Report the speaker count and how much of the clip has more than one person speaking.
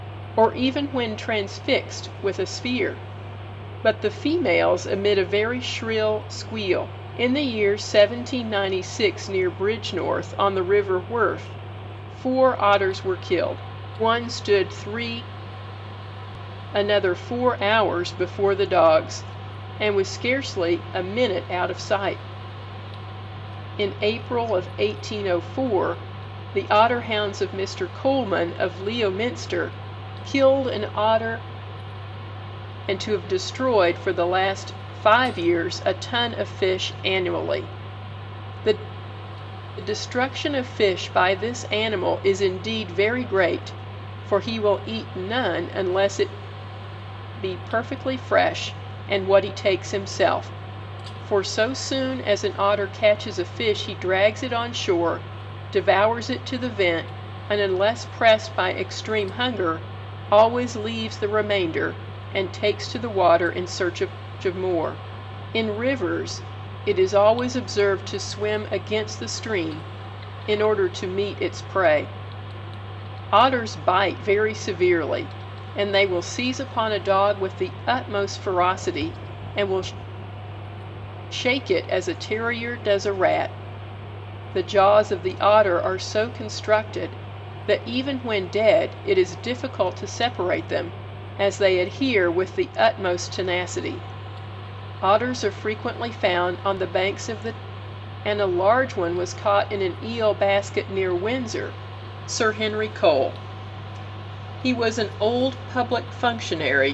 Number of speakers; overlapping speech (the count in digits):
1, no overlap